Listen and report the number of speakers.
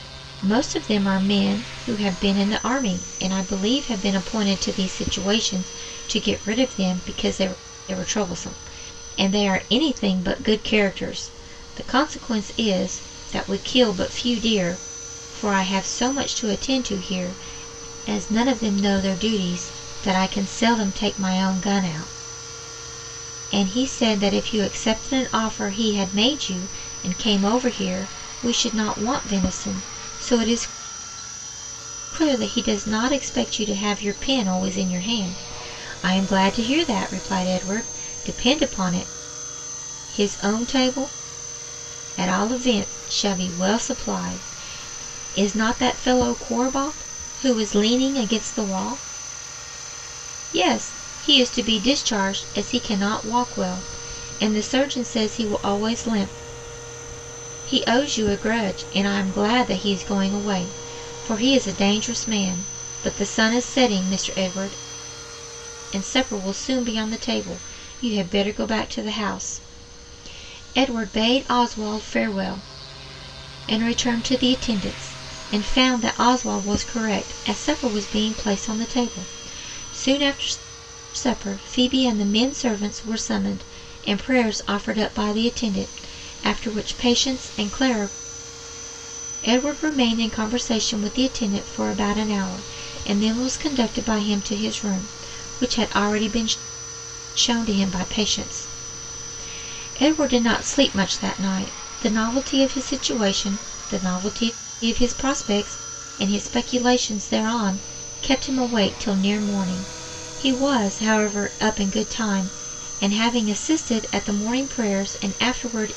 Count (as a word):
one